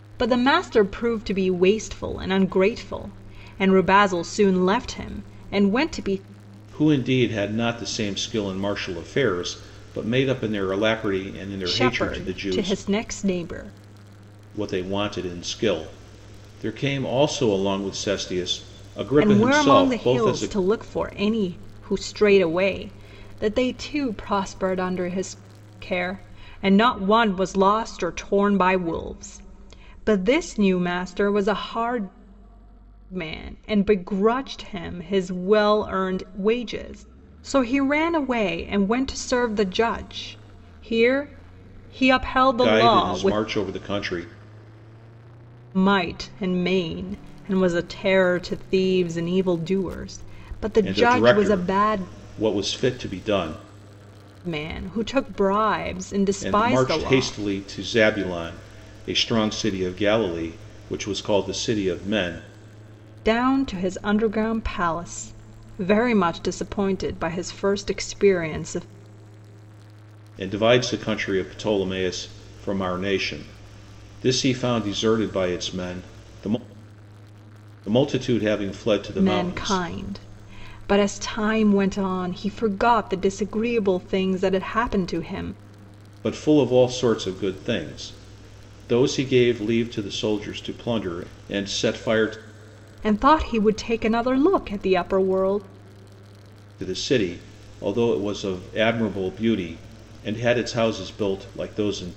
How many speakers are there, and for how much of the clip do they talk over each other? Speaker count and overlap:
two, about 6%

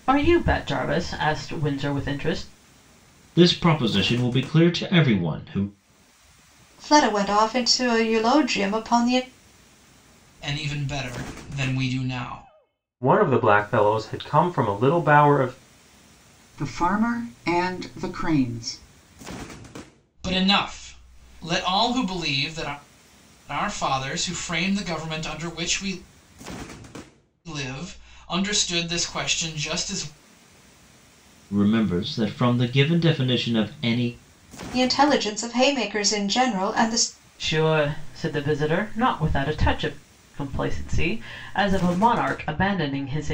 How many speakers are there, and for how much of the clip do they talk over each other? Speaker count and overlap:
six, no overlap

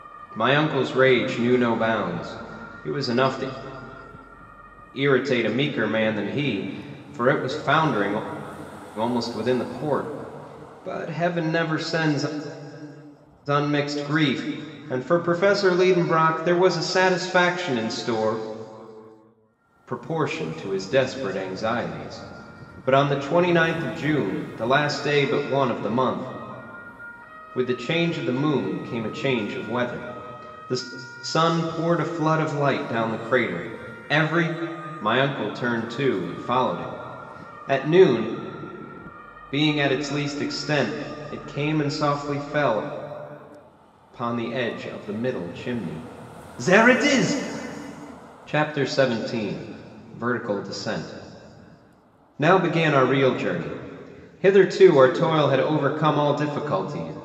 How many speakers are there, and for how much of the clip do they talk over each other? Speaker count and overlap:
one, no overlap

